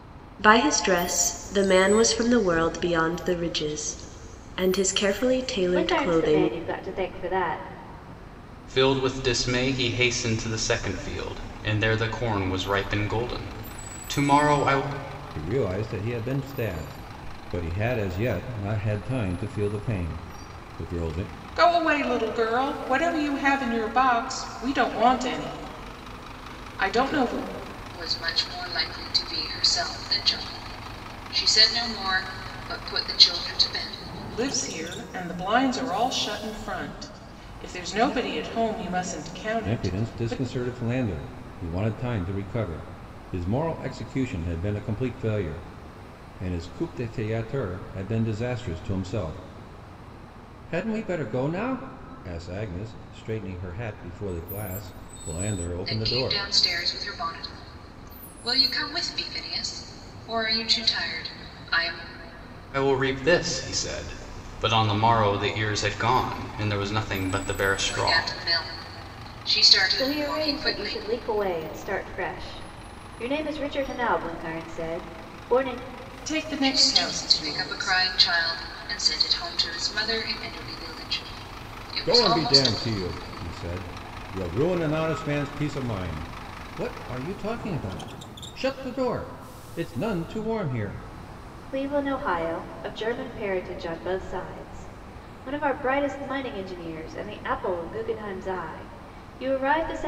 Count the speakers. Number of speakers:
6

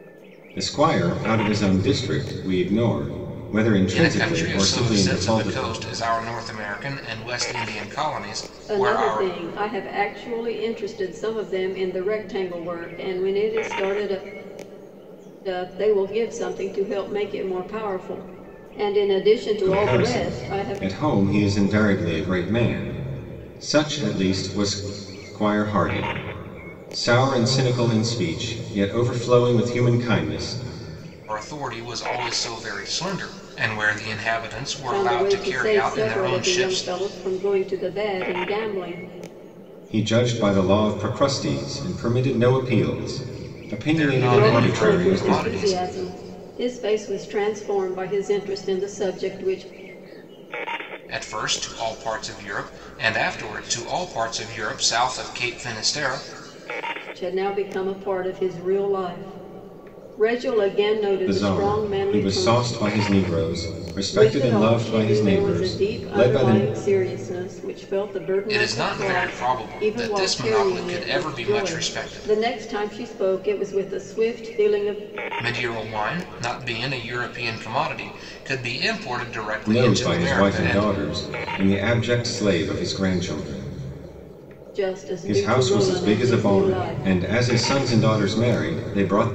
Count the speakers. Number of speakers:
3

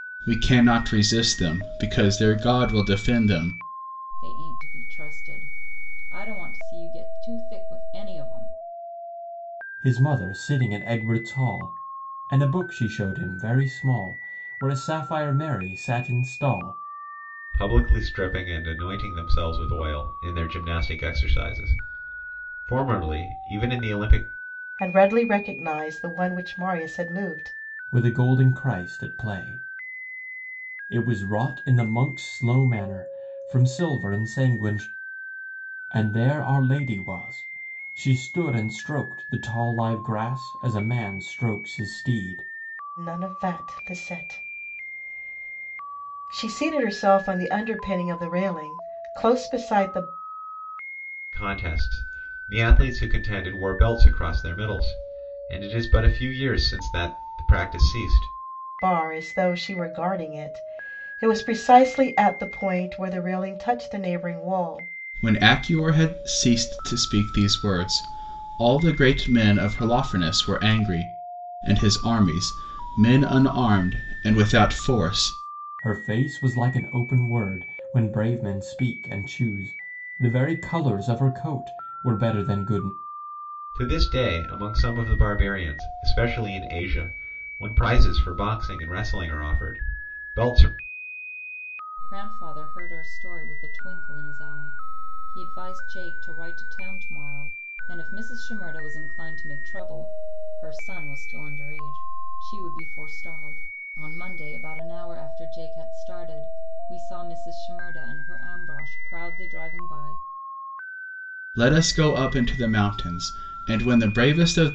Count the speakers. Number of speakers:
5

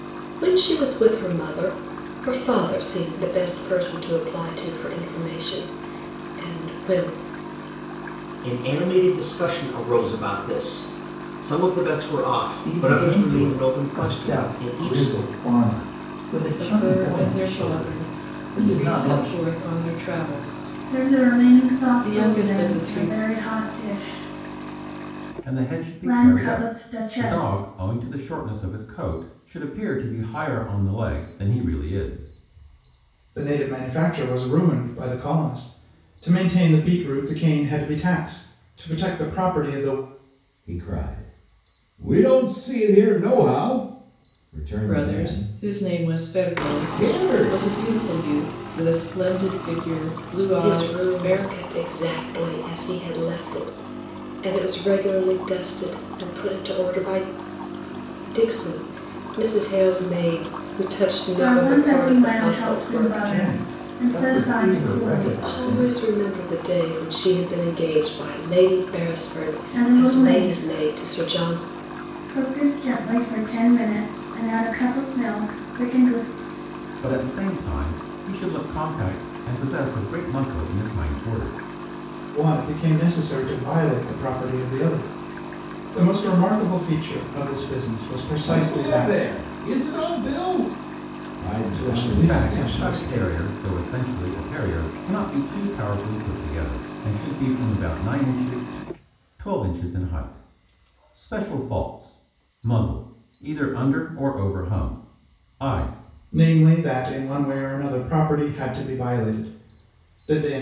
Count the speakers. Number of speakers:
8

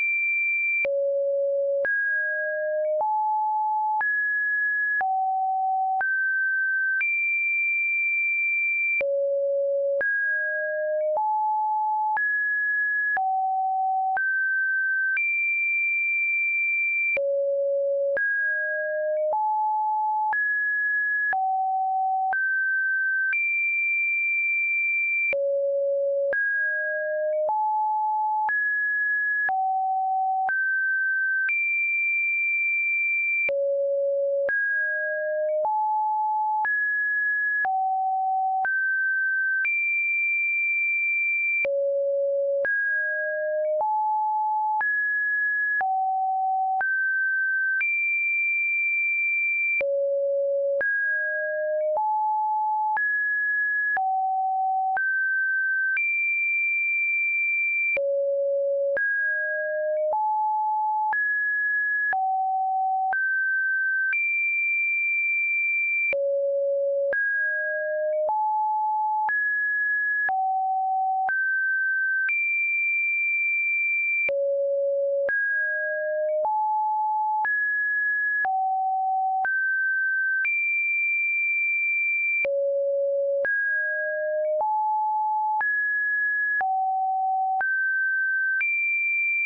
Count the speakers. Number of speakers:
0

